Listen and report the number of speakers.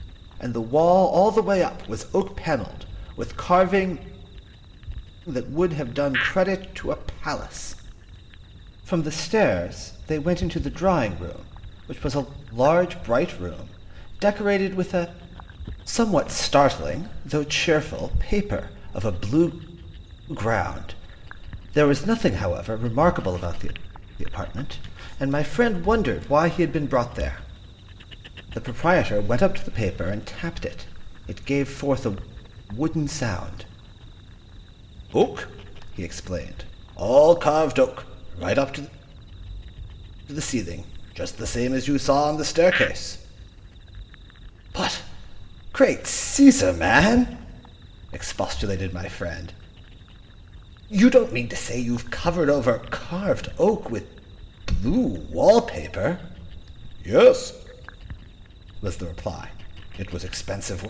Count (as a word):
one